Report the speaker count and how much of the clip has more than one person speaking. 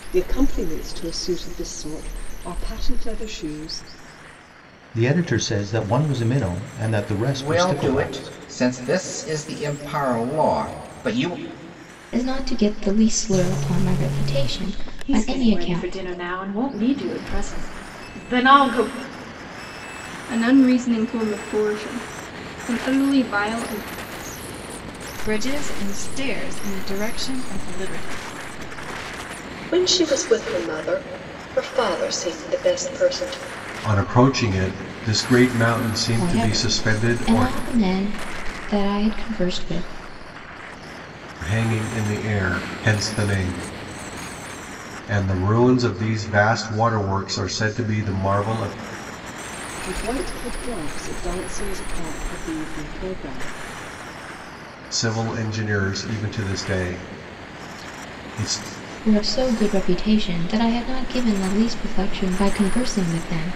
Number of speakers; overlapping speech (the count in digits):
9, about 5%